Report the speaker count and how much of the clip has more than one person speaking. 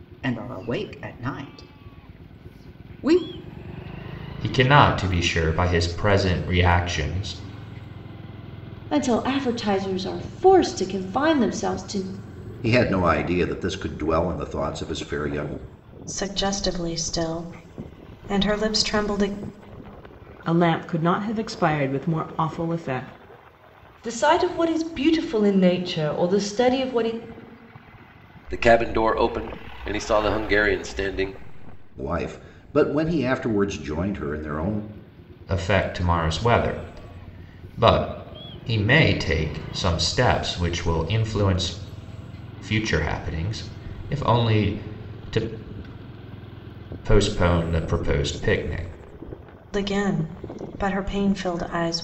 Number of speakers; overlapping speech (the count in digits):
8, no overlap